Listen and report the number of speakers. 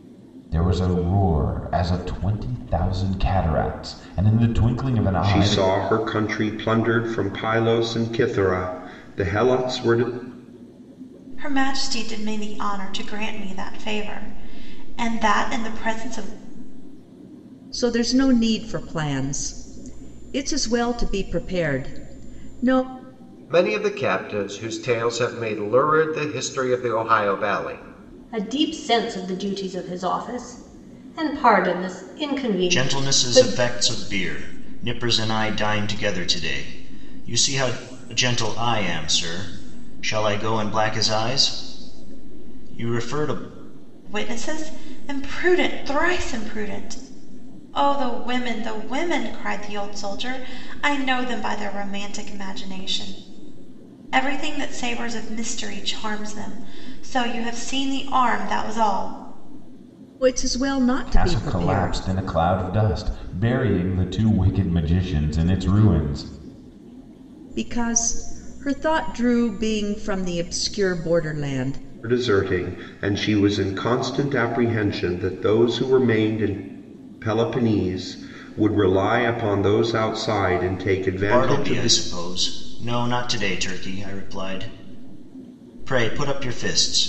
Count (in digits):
7